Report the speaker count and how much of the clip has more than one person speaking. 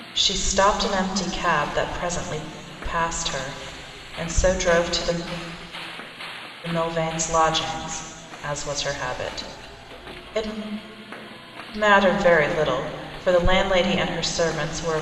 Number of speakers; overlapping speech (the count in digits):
1, no overlap